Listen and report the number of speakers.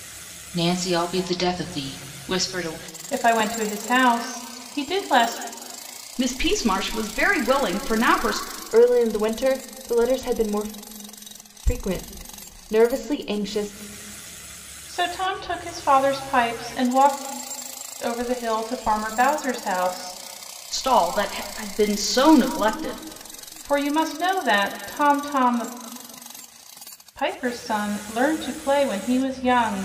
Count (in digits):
4